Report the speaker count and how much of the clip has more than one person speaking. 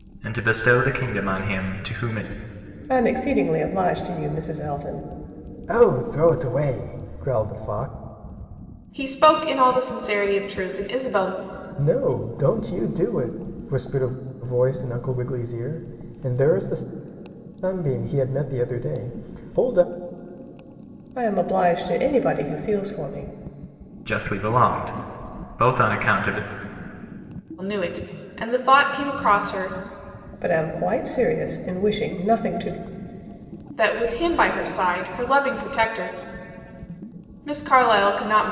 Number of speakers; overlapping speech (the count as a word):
four, no overlap